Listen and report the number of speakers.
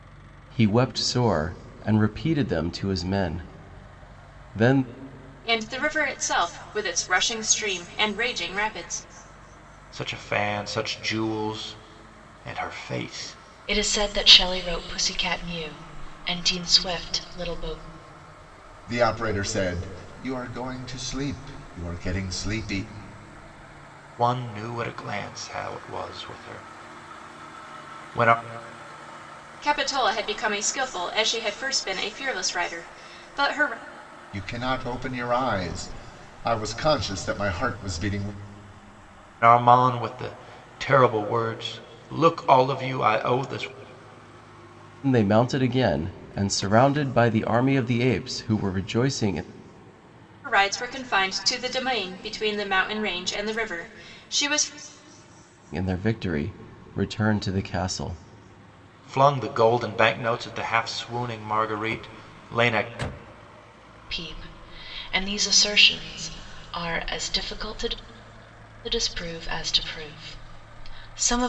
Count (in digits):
5